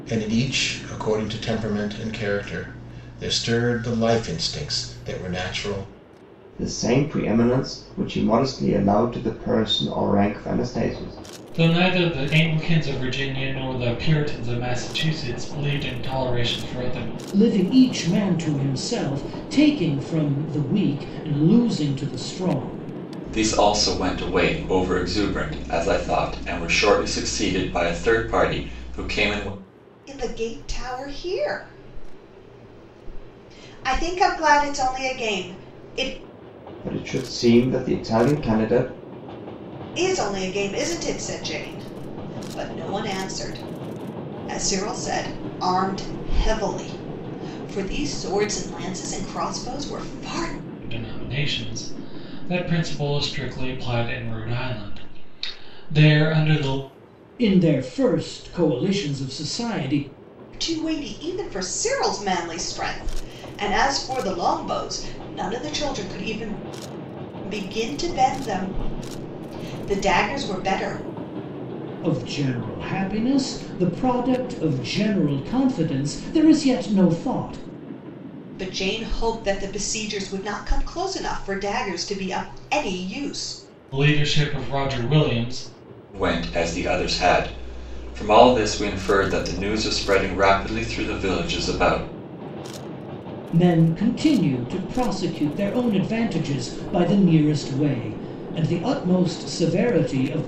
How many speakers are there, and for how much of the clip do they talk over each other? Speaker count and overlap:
6, no overlap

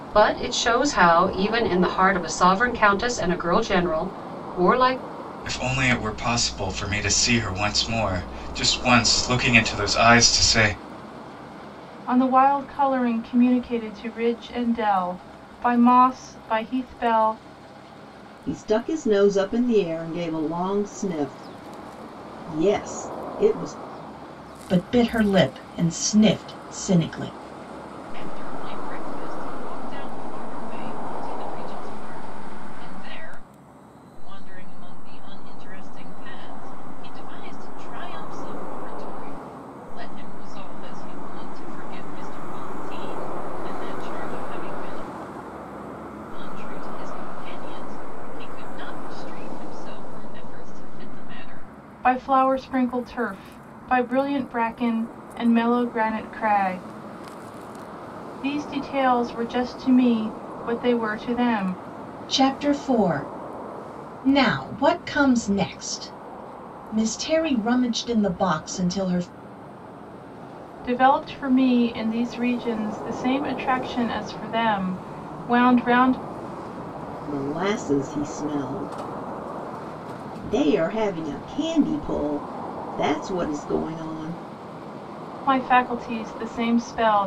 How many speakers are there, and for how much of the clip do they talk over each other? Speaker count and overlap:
6, no overlap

